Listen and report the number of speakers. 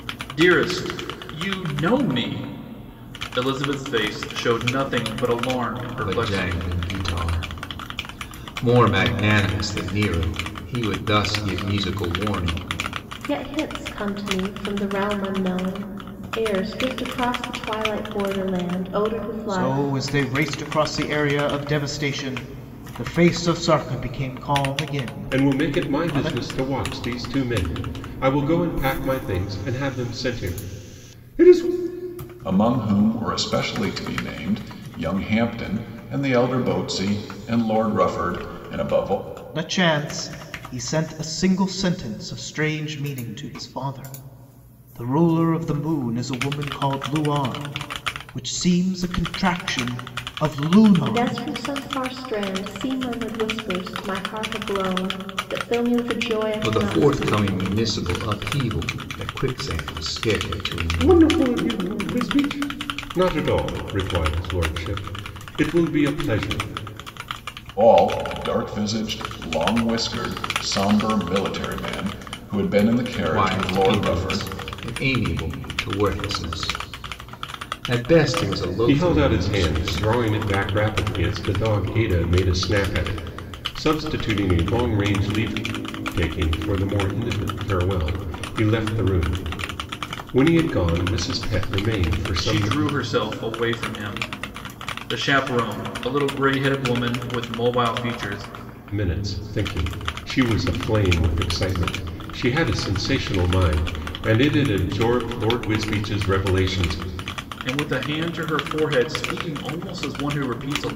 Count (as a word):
six